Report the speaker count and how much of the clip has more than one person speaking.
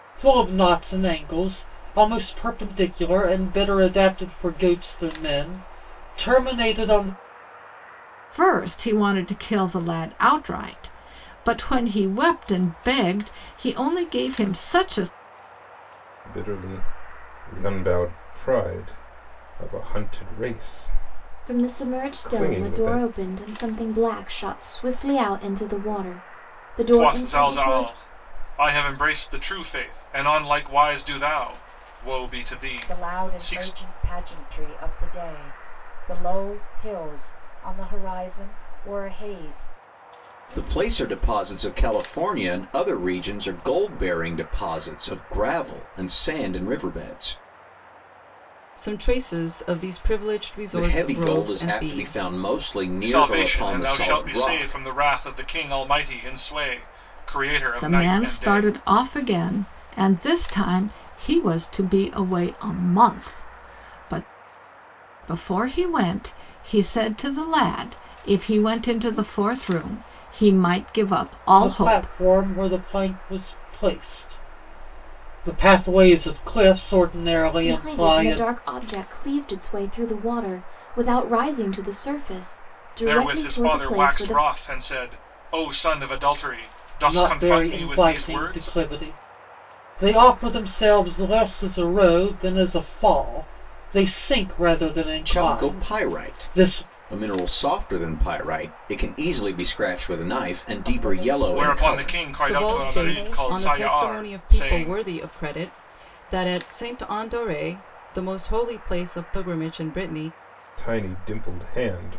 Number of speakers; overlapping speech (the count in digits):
8, about 17%